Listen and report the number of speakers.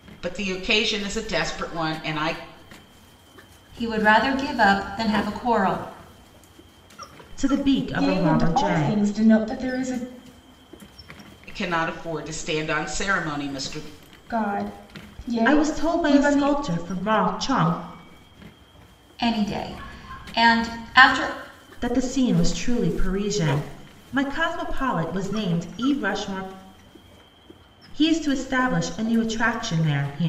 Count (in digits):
4